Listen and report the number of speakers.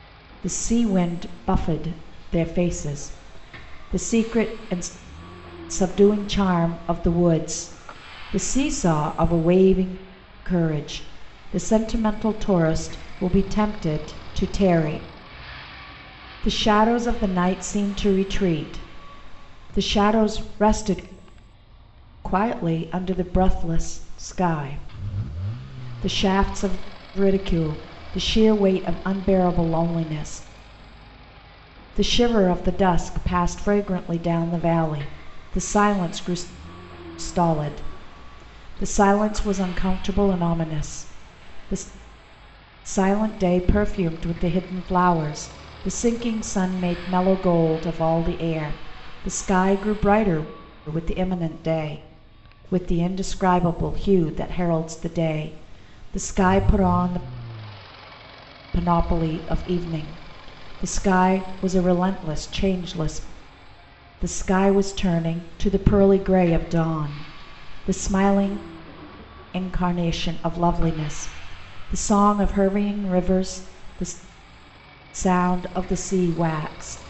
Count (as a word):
one